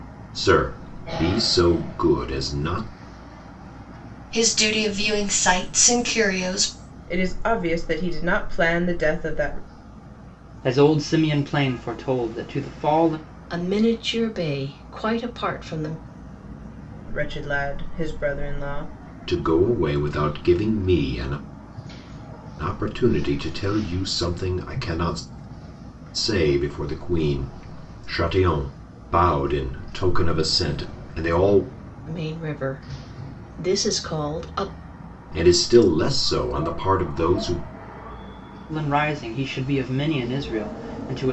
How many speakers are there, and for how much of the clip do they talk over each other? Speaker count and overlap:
5, no overlap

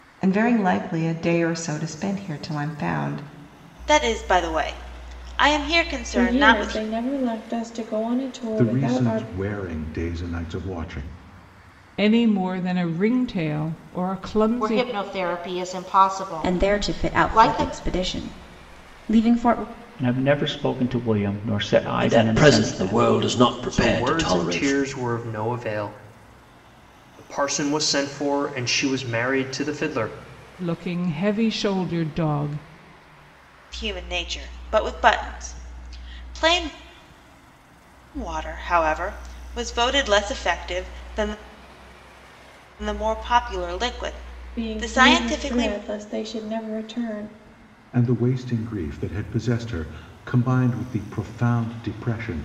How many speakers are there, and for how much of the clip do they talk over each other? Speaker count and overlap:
10, about 13%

